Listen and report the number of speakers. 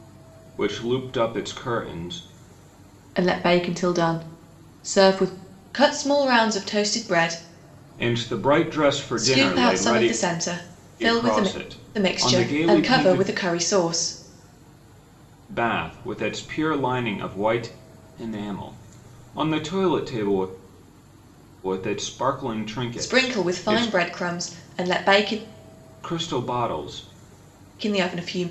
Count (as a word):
two